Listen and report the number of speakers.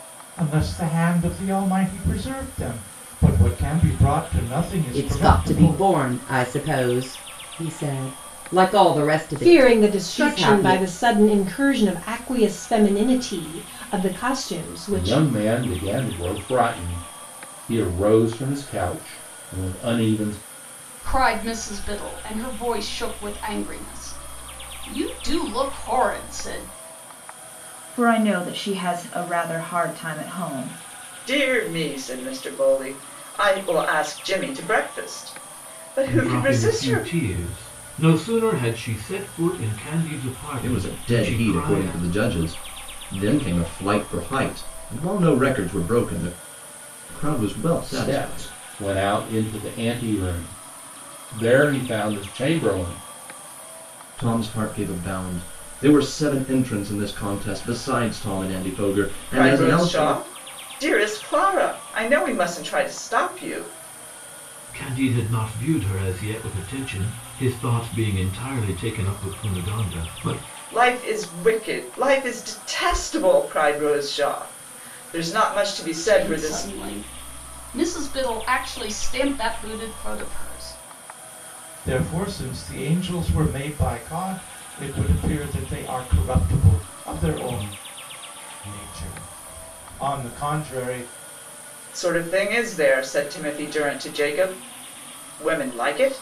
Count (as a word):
nine